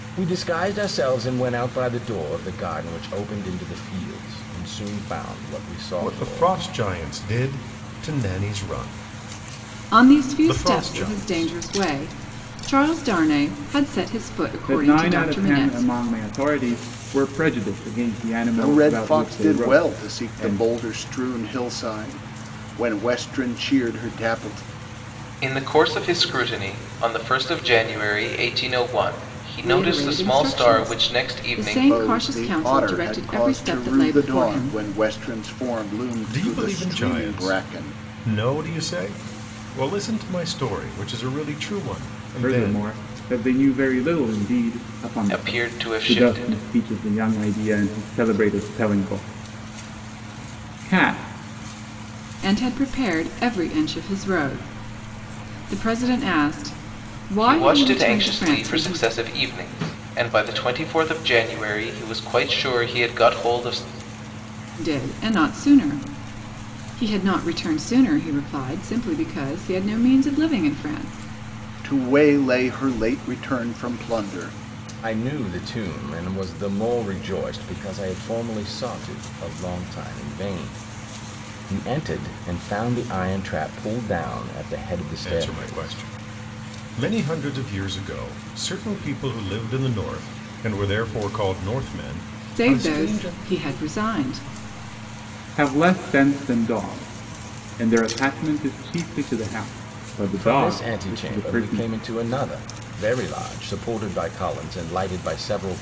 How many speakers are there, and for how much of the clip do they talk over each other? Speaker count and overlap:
six, about 18%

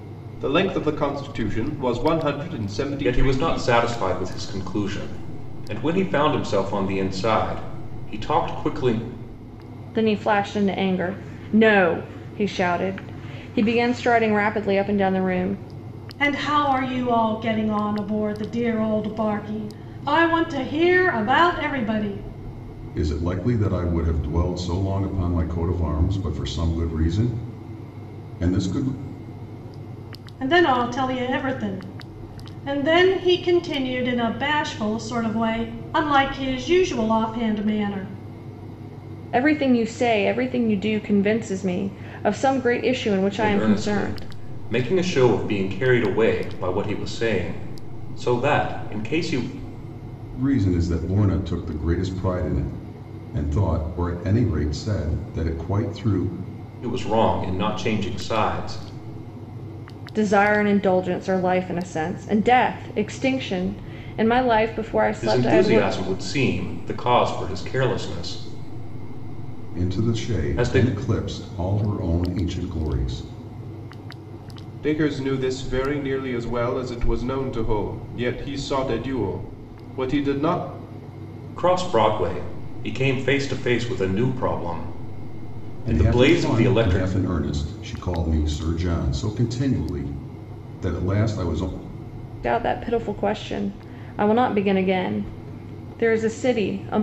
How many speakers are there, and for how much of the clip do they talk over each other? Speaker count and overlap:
five, about 5%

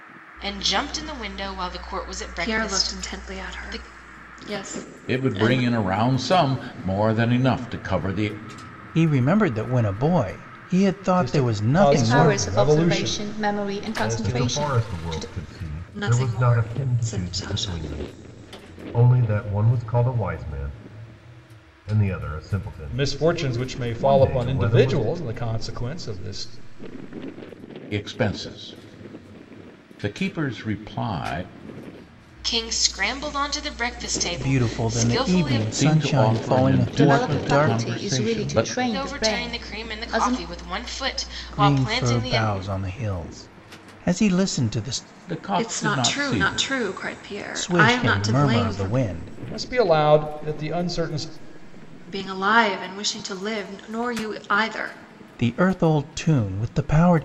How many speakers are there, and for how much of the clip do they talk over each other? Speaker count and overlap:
seven, about 35%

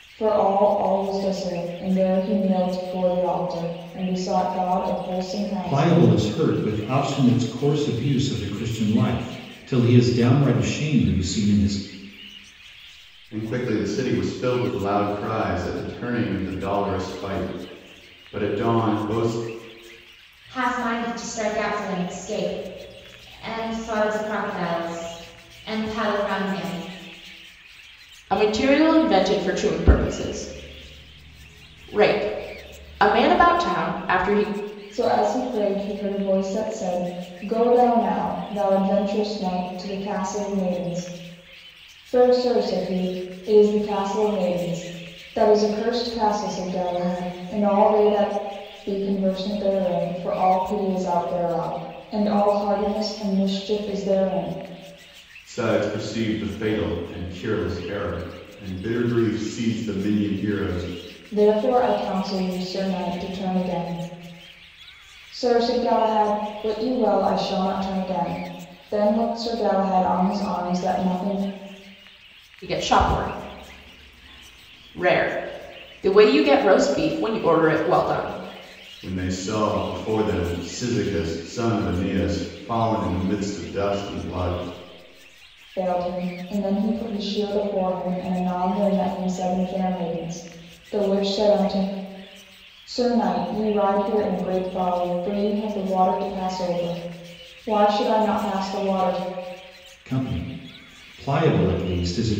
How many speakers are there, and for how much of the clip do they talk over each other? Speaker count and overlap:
five, under 1%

